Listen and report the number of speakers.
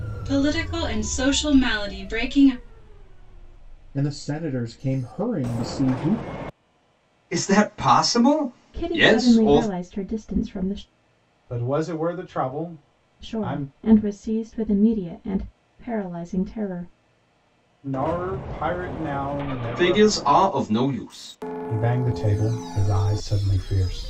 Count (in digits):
5